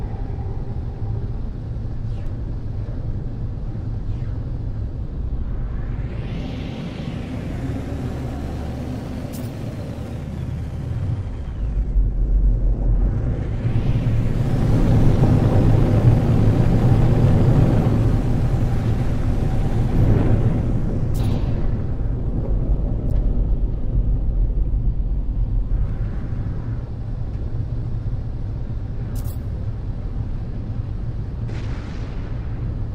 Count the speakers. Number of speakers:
zero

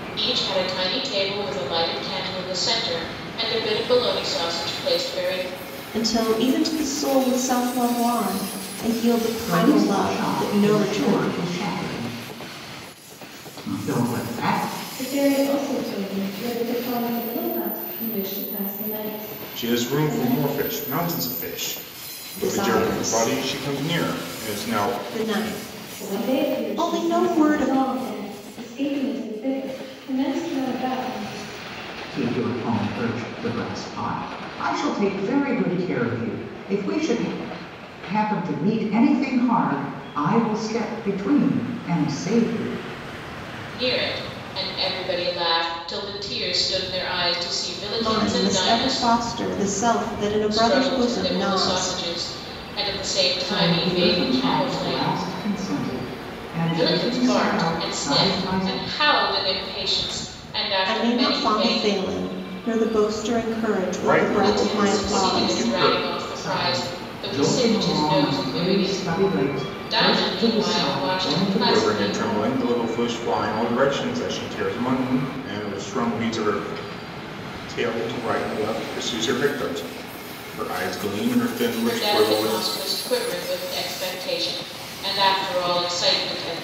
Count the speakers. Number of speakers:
five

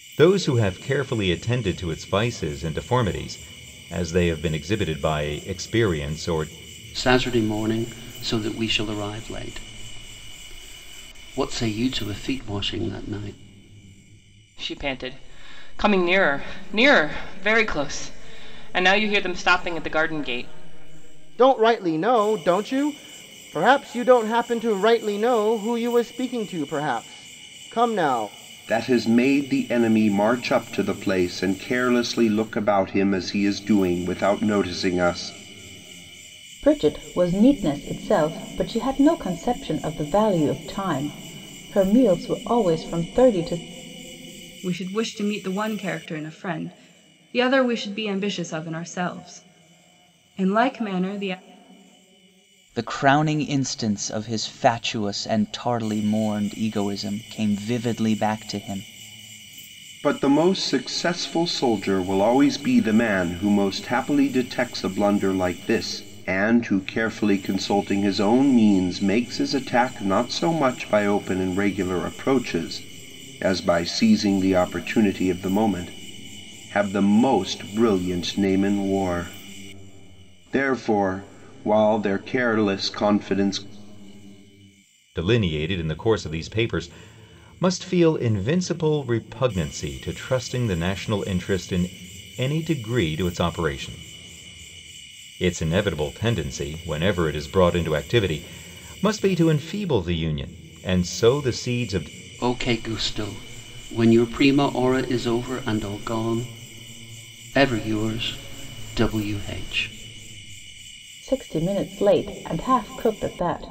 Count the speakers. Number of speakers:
eight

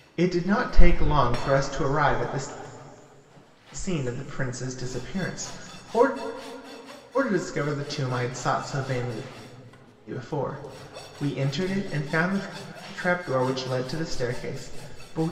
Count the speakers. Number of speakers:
one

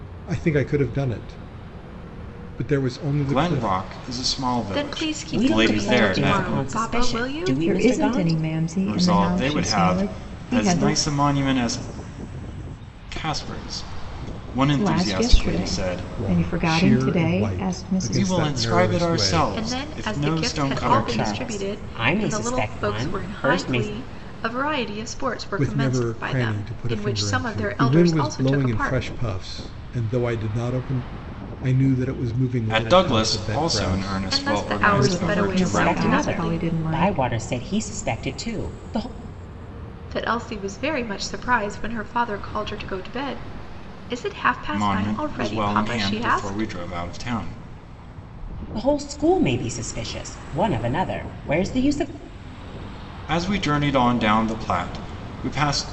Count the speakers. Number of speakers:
five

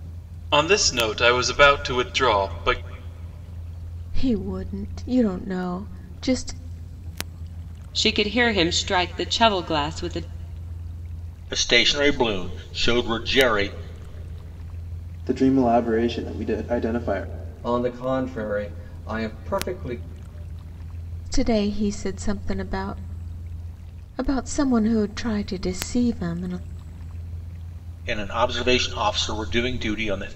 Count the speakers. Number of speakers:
six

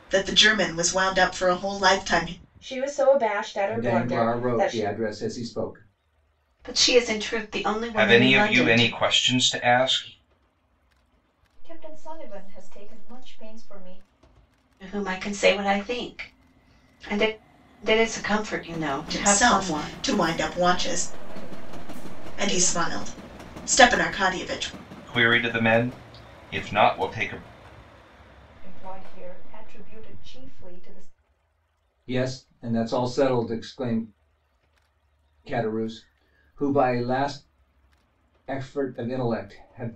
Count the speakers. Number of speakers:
six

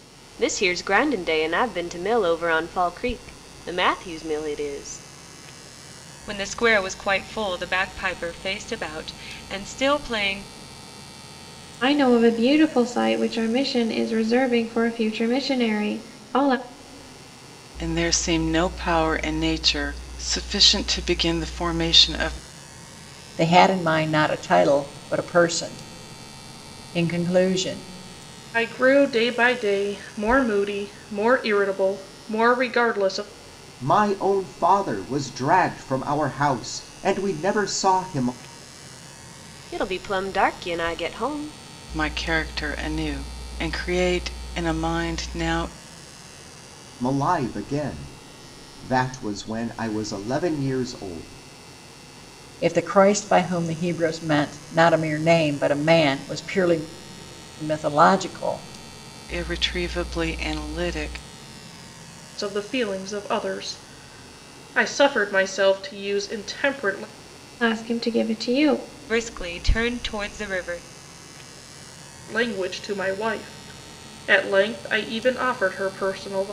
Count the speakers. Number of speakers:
seven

